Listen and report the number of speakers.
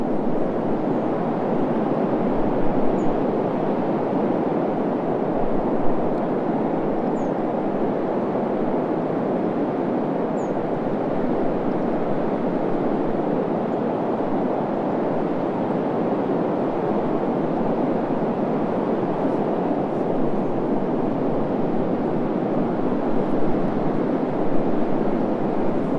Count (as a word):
zero